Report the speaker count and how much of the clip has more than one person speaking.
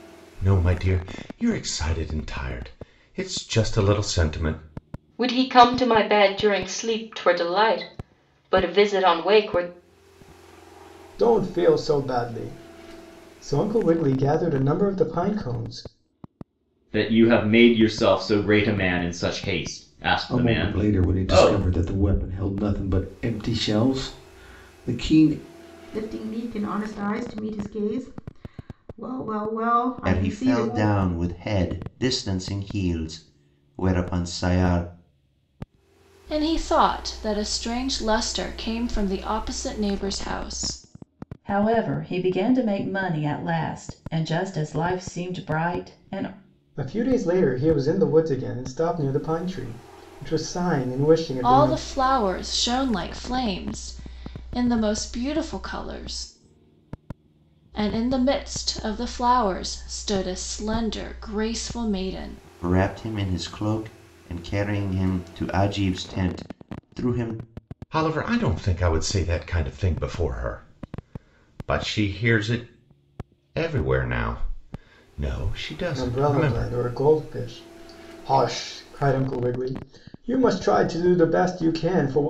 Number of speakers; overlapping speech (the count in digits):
9, about 4%